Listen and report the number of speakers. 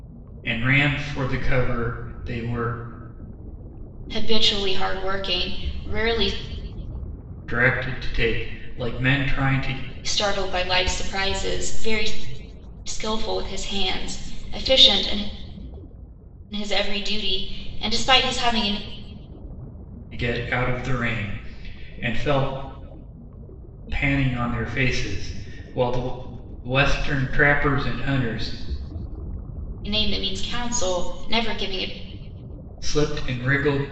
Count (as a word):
two